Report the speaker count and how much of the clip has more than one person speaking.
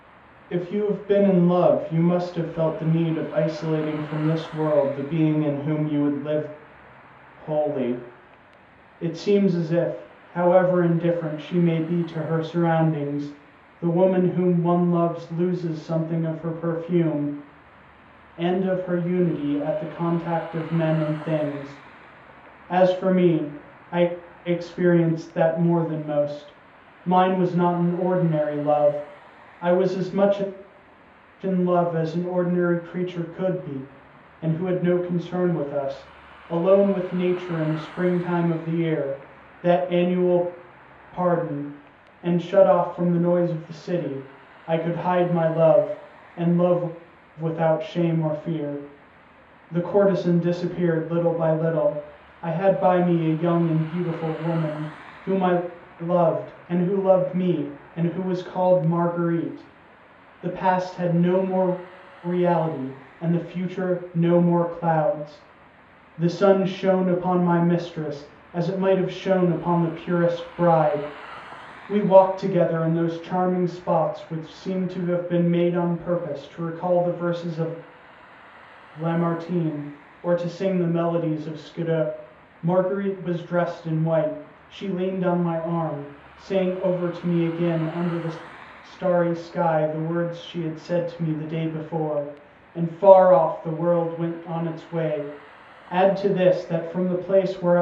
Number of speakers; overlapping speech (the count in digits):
1, no overlap